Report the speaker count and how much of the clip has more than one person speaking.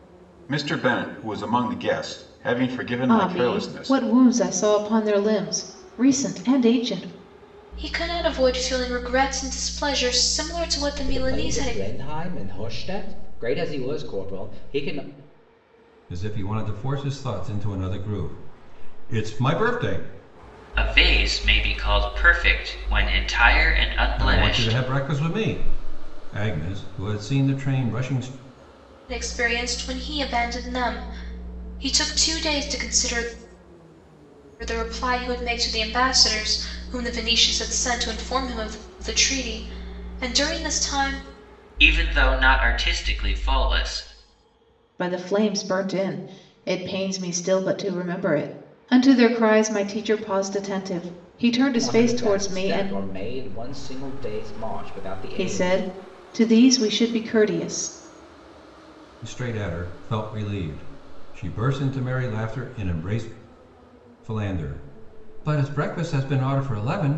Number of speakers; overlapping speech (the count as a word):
six, about 6%